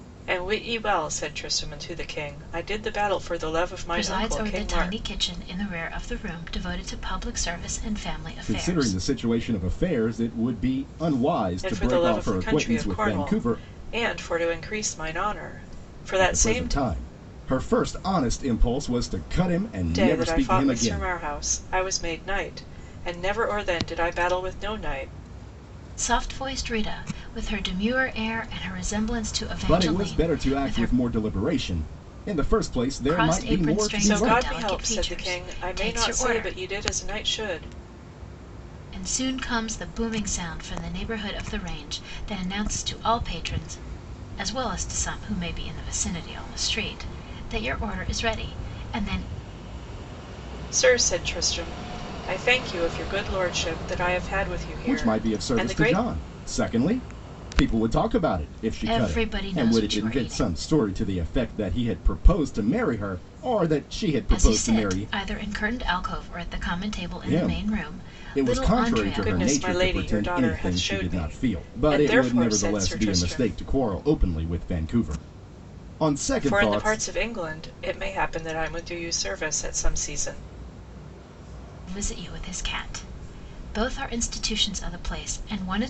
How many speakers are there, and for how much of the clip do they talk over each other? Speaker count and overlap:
three, about 25%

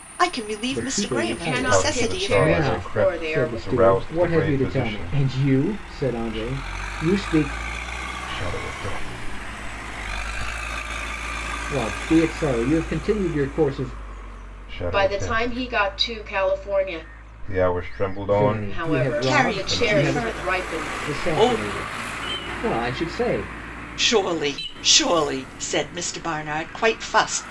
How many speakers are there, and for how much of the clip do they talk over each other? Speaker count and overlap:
four, about 35%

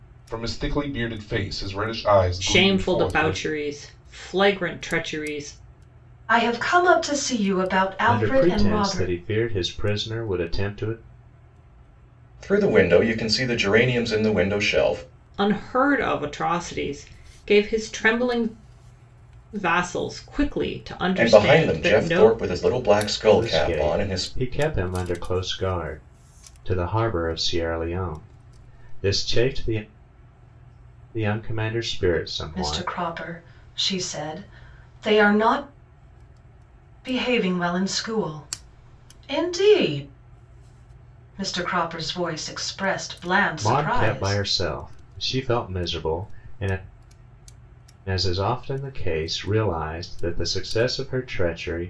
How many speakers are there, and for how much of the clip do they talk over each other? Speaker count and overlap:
five, about 11%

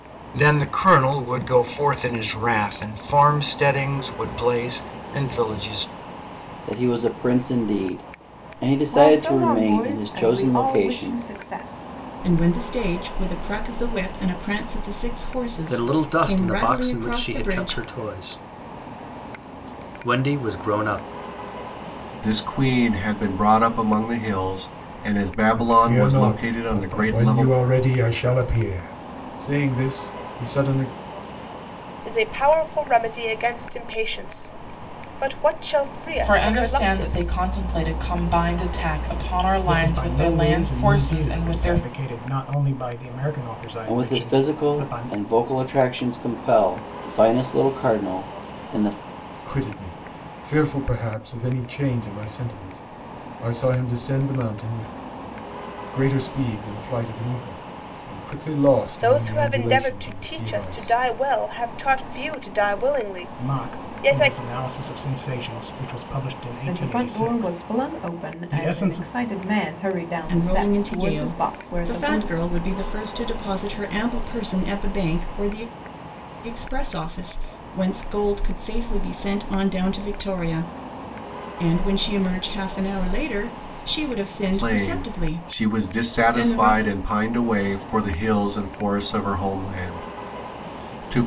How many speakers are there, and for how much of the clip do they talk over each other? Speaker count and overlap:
ten, about 24%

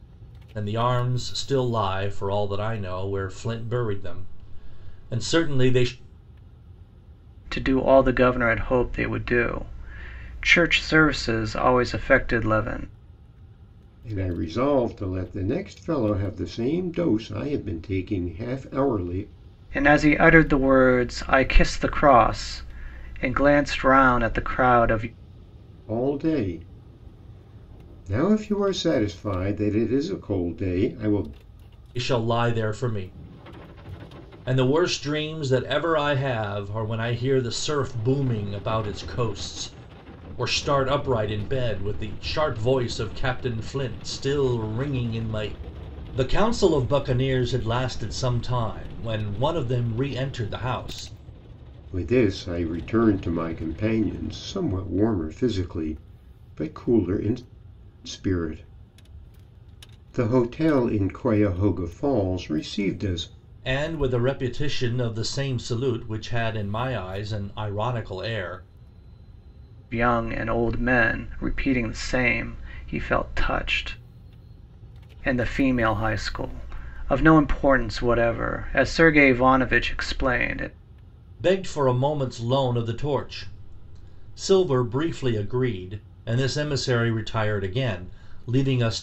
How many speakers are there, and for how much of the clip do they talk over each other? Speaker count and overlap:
three, no overlap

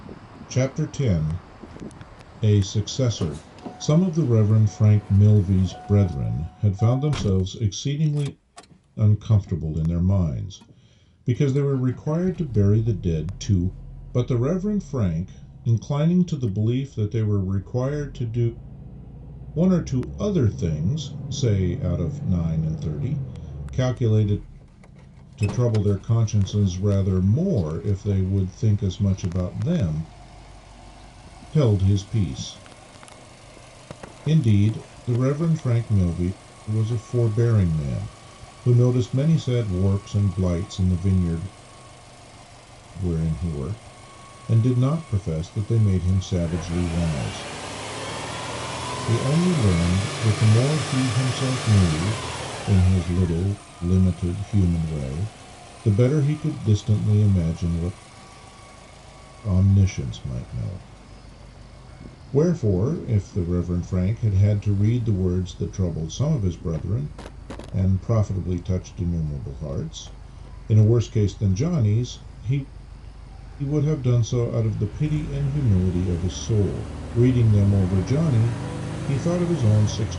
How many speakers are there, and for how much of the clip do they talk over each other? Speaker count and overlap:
one, no overlap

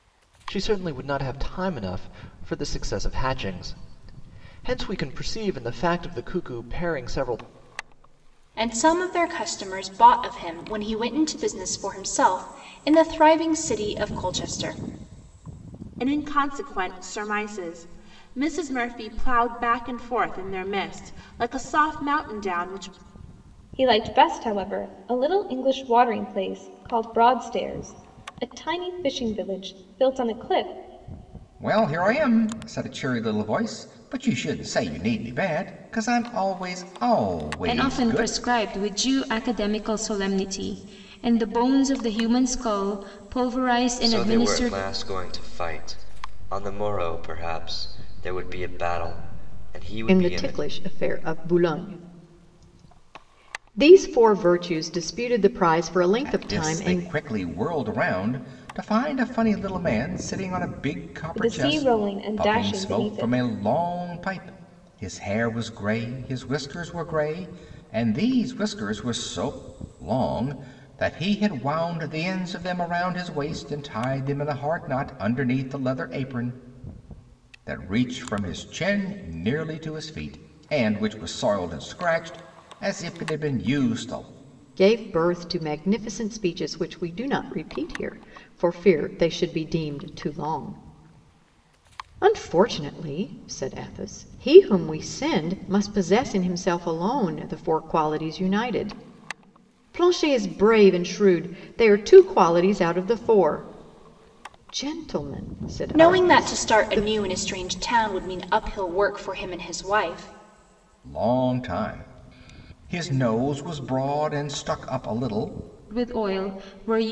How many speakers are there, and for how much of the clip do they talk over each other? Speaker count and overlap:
eight, about 5%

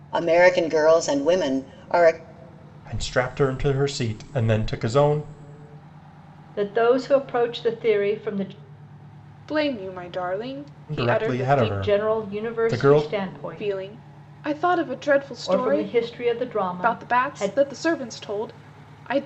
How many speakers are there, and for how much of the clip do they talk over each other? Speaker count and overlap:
four, about 20%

